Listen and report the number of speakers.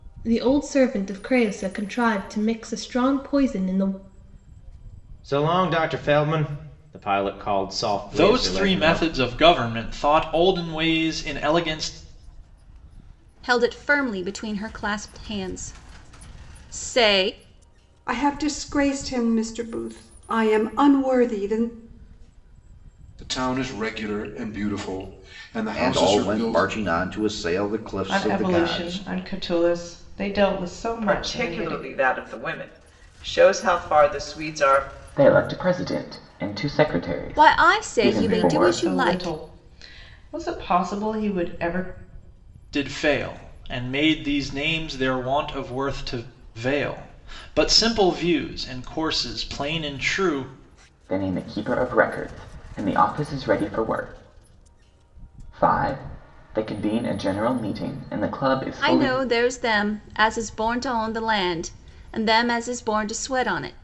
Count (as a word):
ten